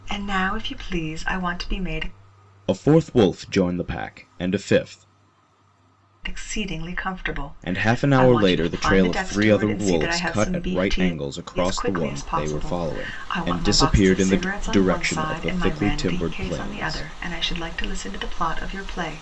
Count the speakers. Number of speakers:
2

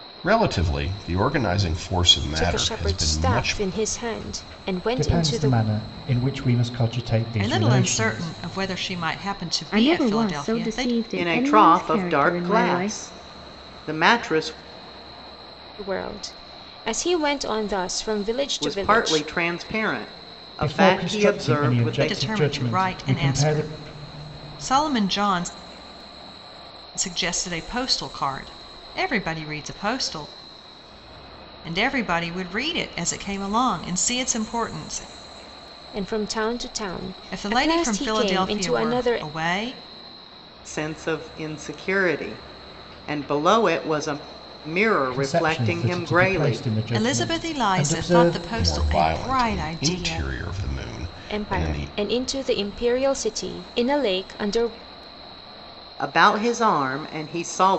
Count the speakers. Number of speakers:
6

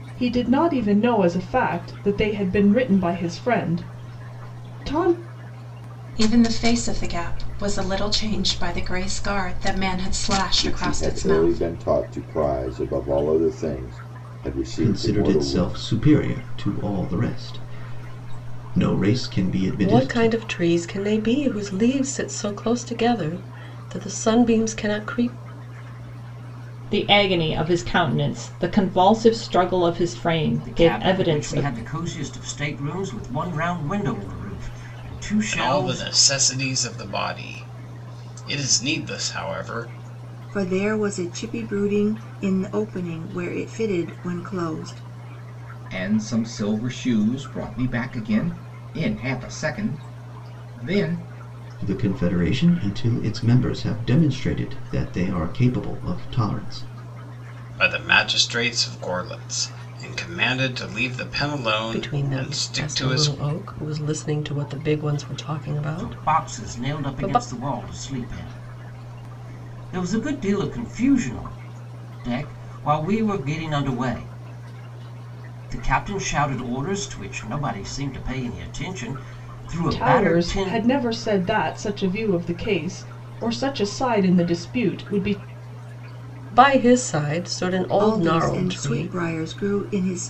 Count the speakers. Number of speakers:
10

